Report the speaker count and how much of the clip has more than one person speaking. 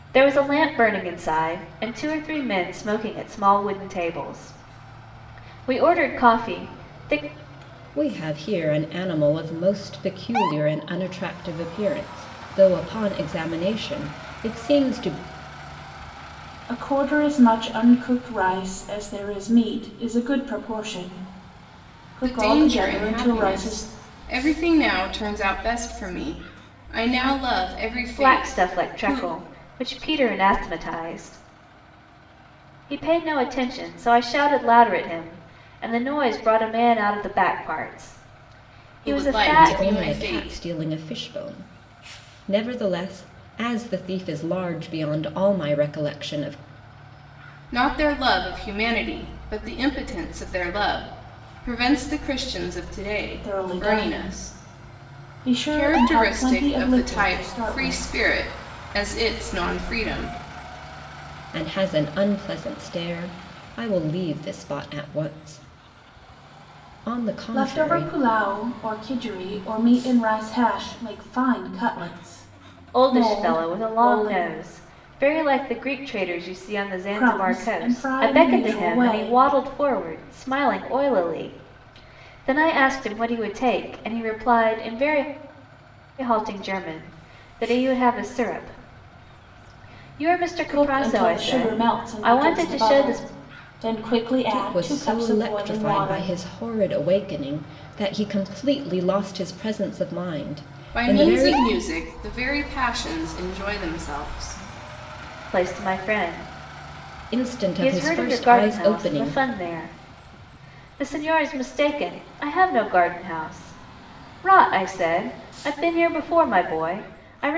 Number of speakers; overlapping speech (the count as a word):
four, about 17%